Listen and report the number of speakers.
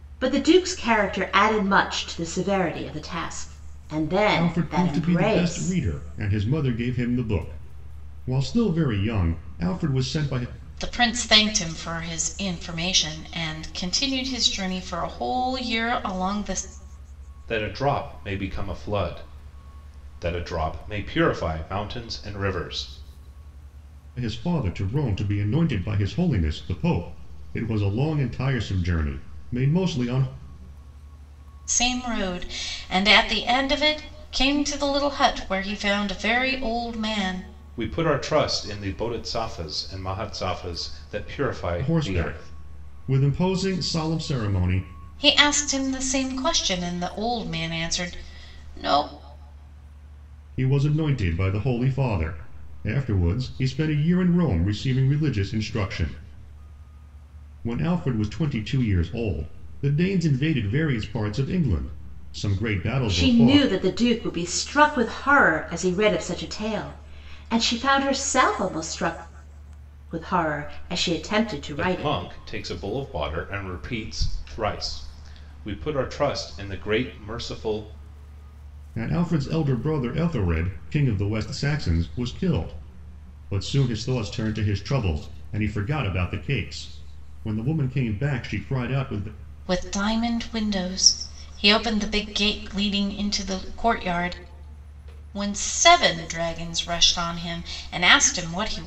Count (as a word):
four